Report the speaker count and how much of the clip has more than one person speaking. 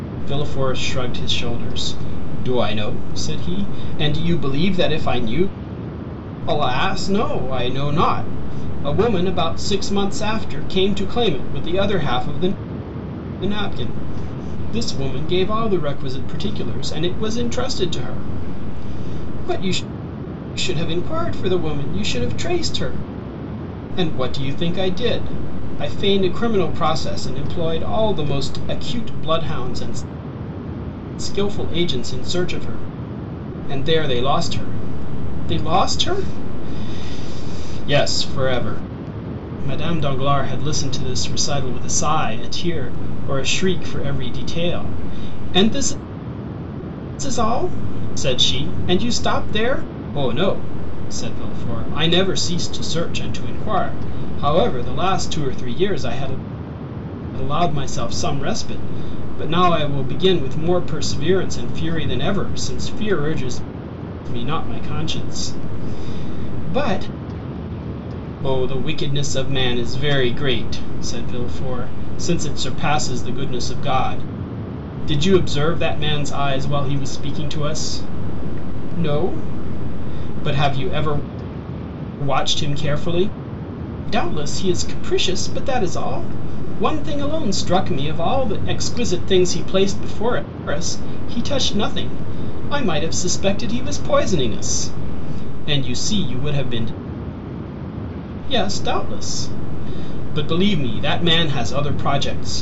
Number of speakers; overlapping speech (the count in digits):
1, no overlap